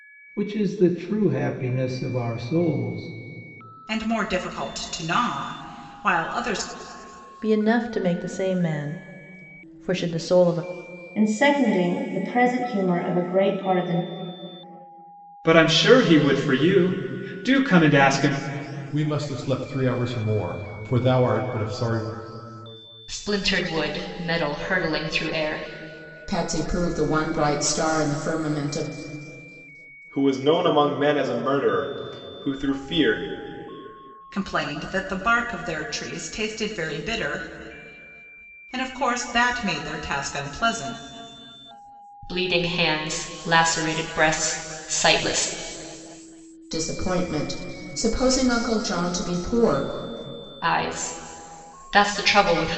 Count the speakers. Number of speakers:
nine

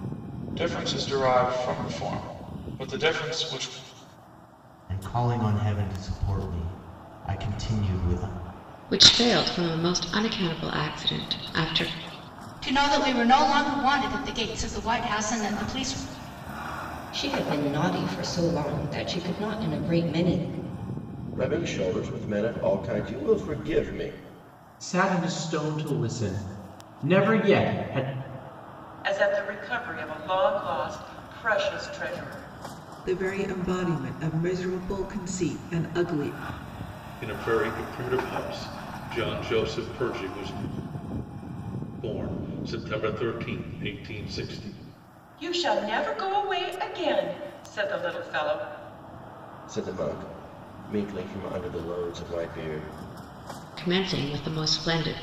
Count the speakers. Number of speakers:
ten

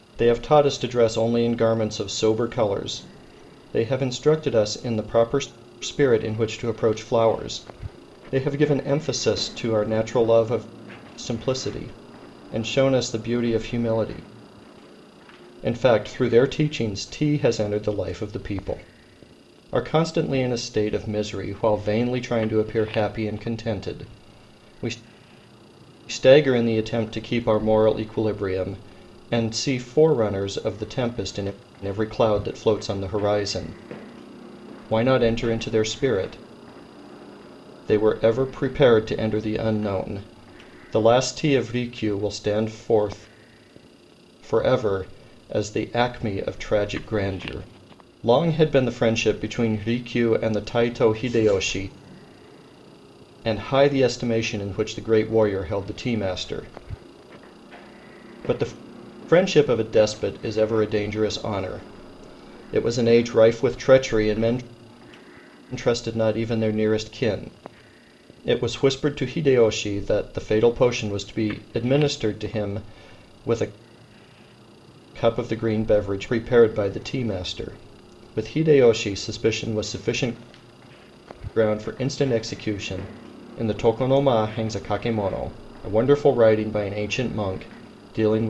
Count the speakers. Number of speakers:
one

